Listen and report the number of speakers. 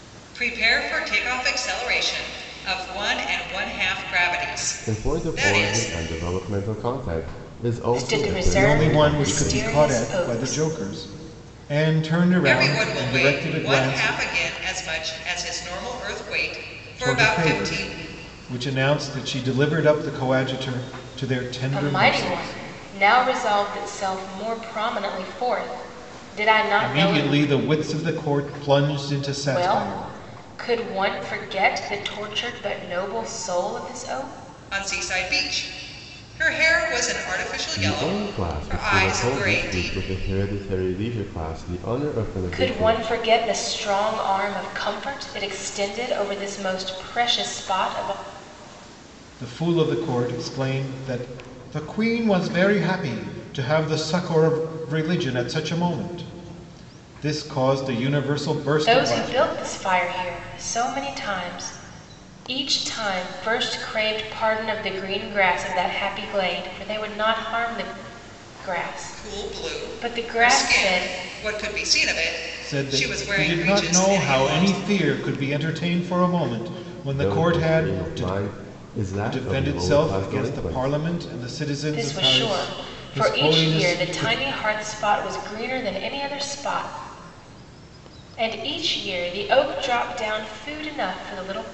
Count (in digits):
4